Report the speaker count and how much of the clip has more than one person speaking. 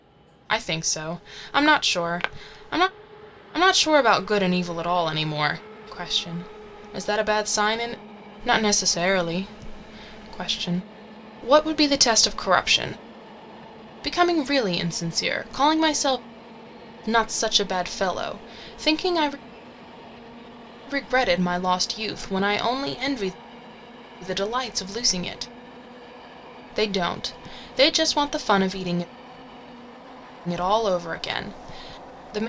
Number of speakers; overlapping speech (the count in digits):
1, no overlap